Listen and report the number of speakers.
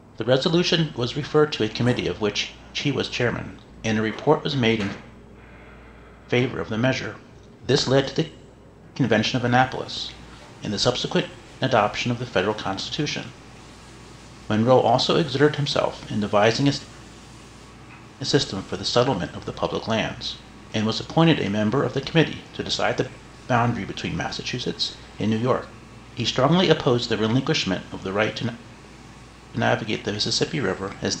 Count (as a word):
one